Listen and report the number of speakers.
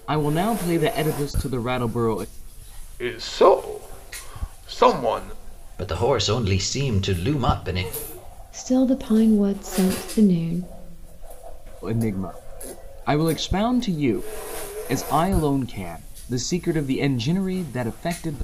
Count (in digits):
4